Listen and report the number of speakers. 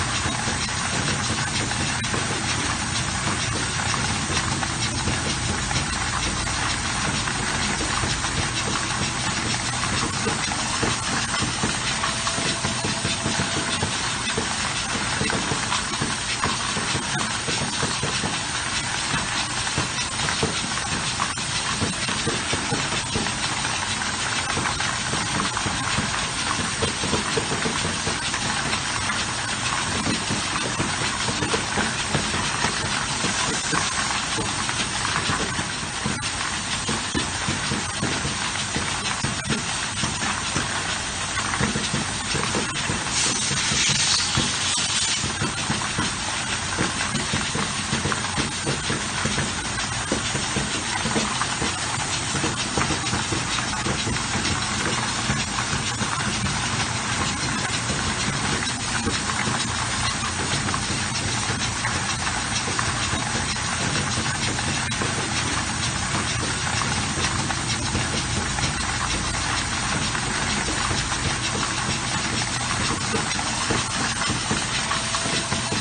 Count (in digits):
0